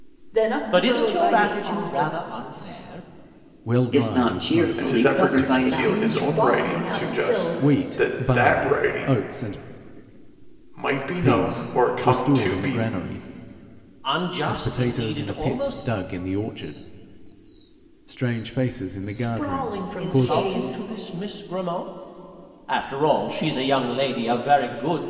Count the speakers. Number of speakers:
five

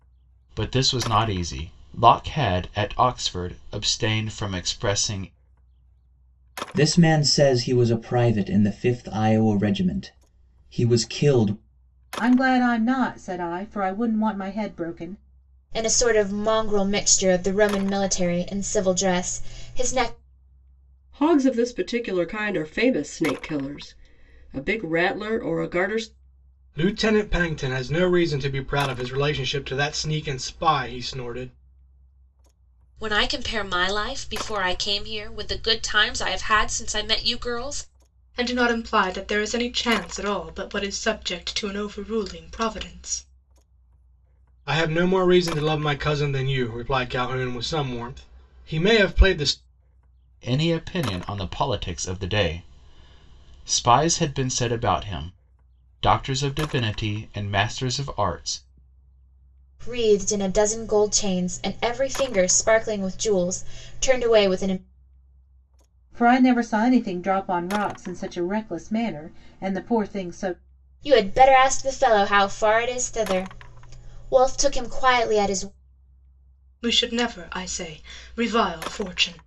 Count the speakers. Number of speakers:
eight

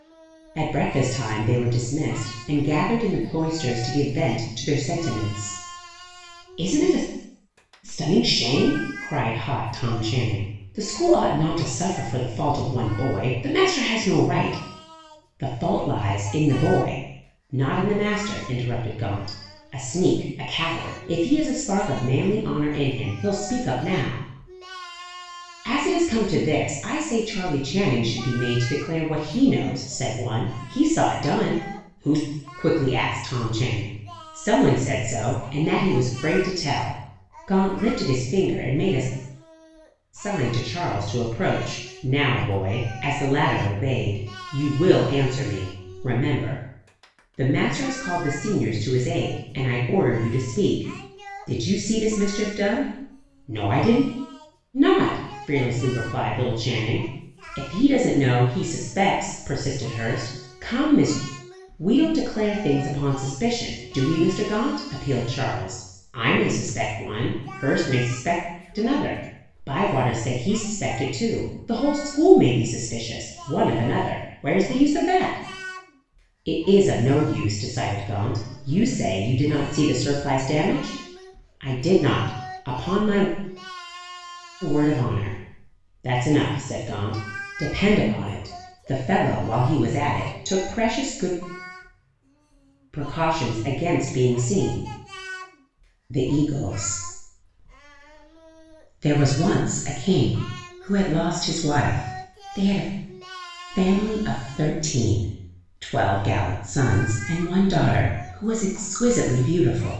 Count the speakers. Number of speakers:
one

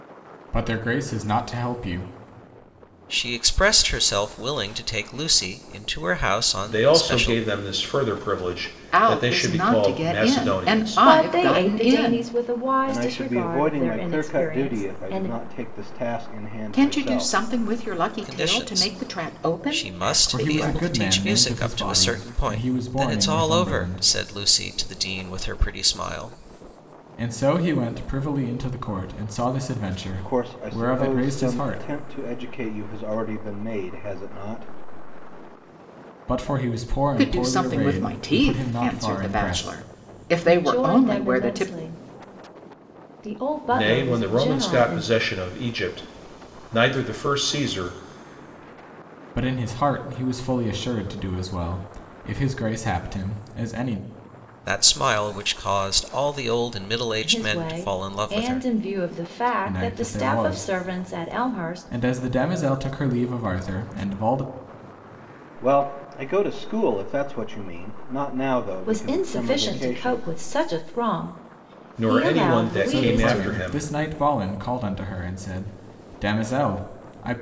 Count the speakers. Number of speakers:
six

